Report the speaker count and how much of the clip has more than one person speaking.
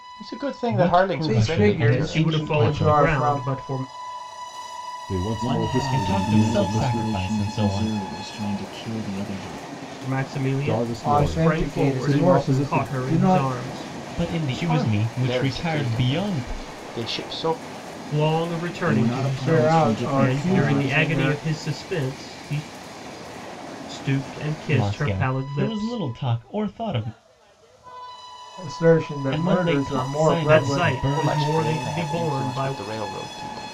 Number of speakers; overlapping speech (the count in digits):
6, about 52%